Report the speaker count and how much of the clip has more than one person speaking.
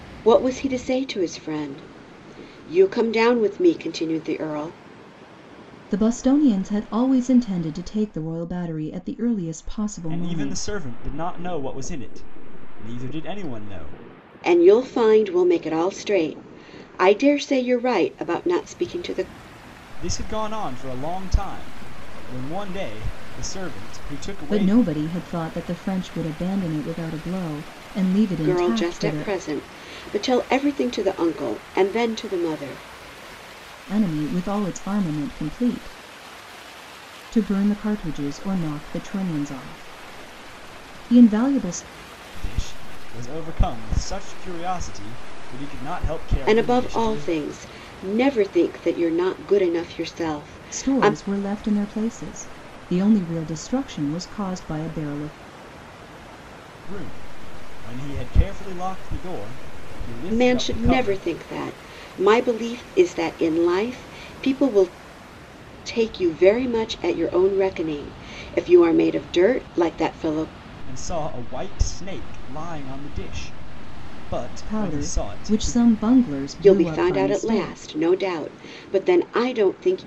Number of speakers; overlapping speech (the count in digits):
3, about 9%